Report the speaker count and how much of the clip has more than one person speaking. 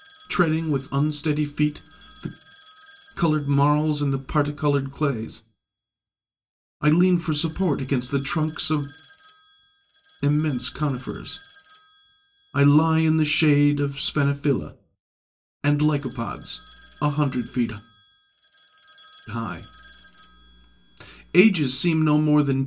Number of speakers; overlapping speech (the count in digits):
1, no overlap